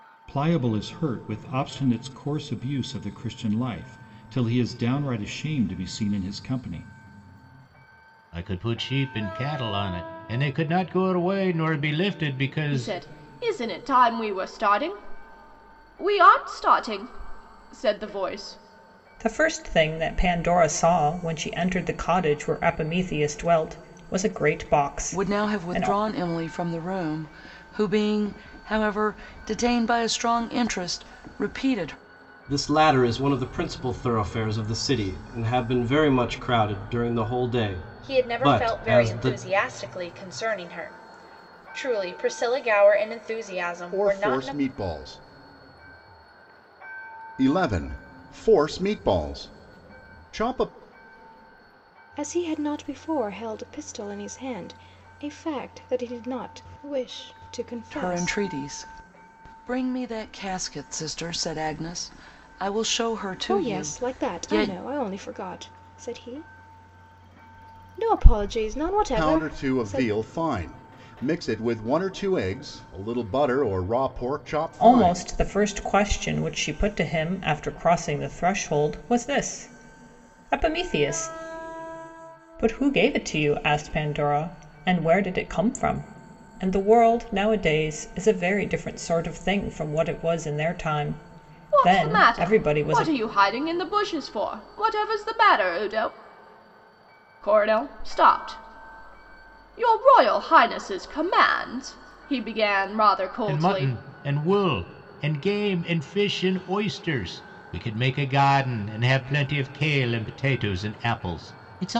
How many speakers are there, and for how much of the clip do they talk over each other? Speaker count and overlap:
nine, about 8%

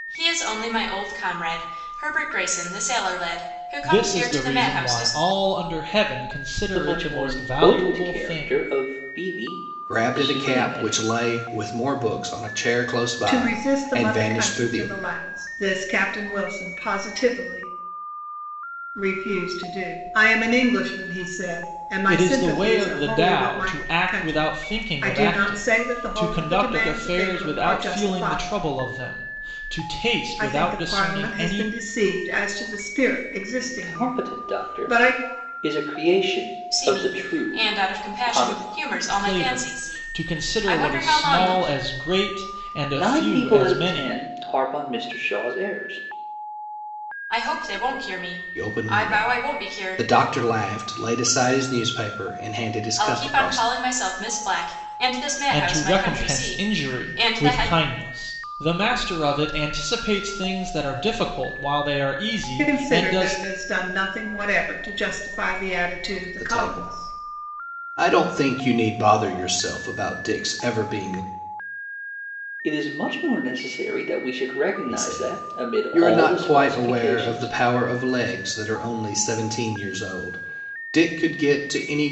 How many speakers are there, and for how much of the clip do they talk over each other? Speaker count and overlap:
five, about 39%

